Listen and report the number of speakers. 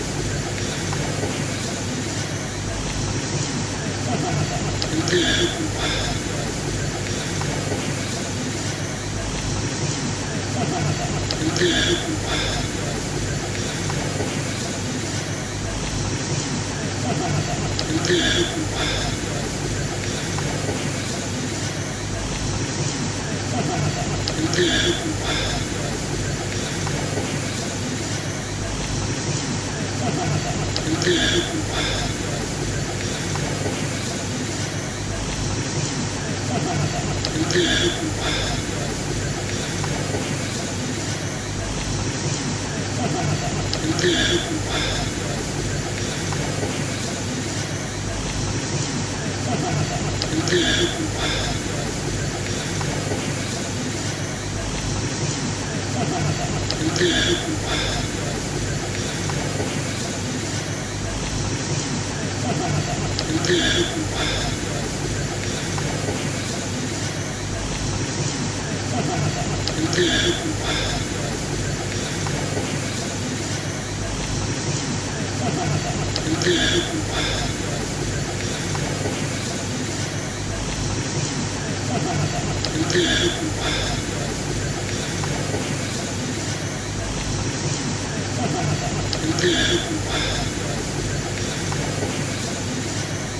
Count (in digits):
0